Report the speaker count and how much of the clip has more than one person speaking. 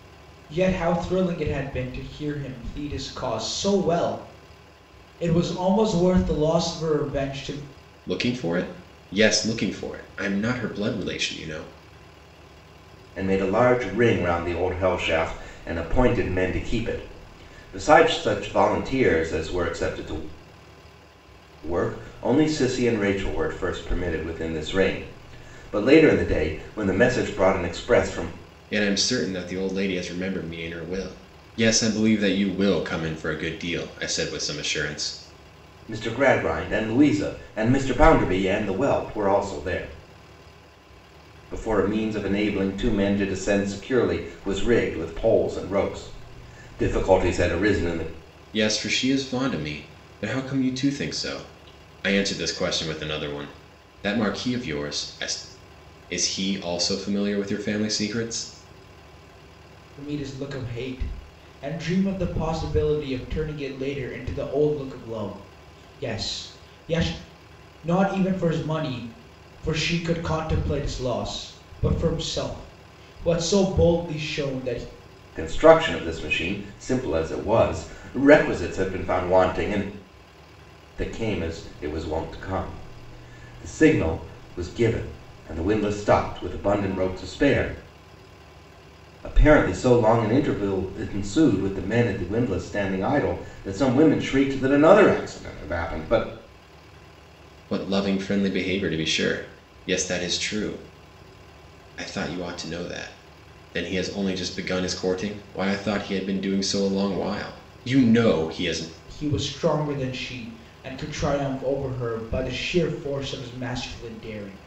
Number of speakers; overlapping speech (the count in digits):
3, no overlap